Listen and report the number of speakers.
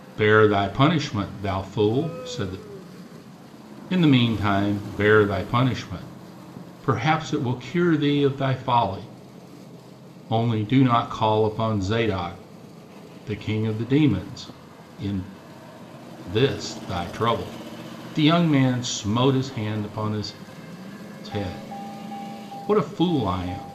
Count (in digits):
1